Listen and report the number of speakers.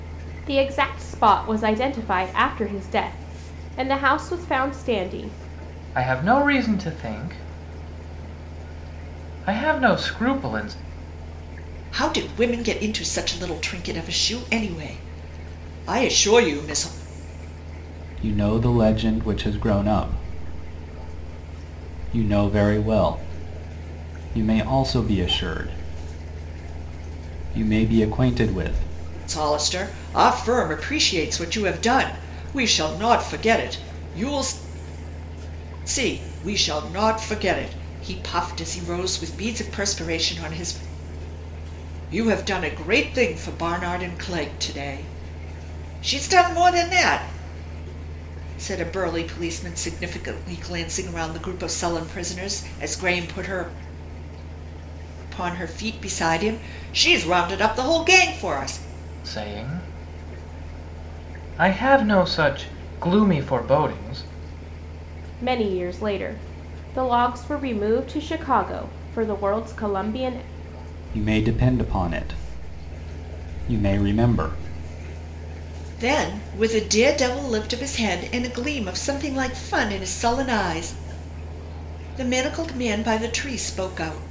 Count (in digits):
4